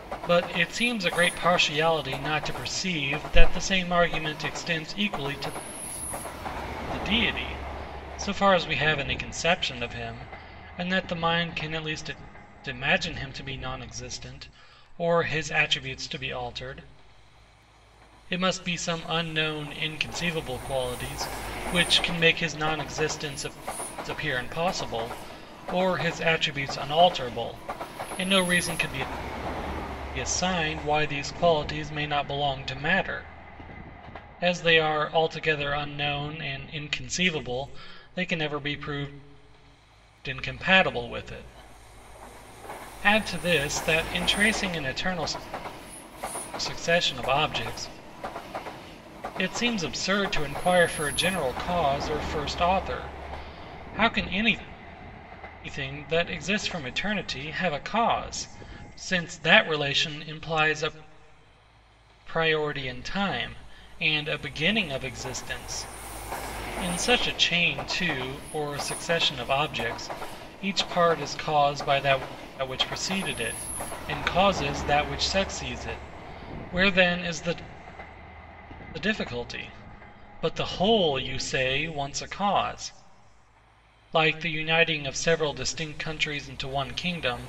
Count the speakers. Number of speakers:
1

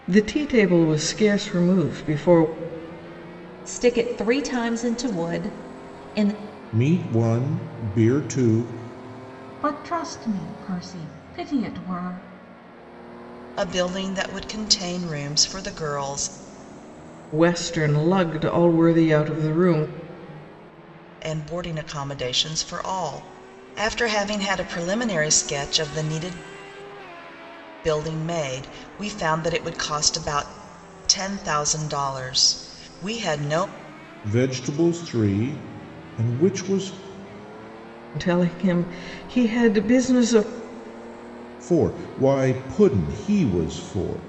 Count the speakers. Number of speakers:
5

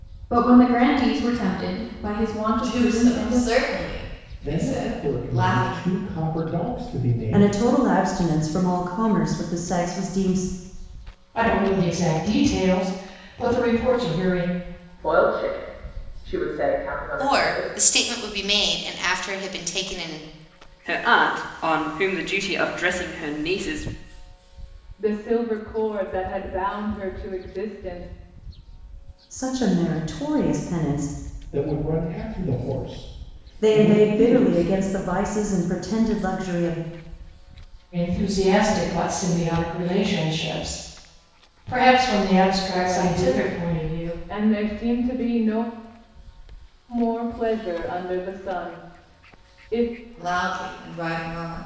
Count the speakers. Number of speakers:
9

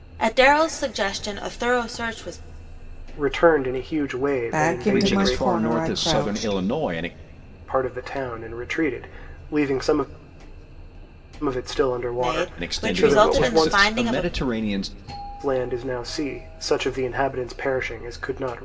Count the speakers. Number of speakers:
4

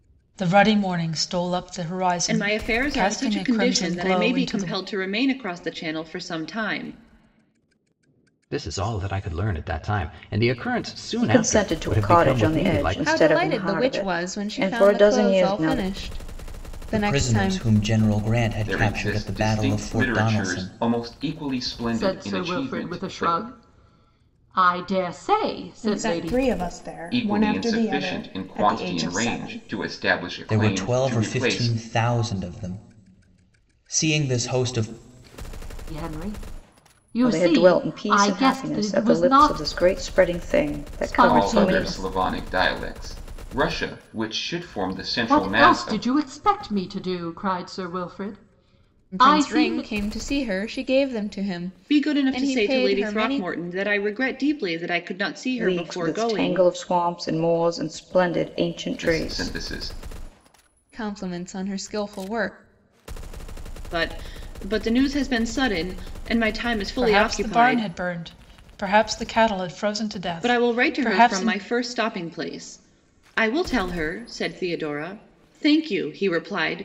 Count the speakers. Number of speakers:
9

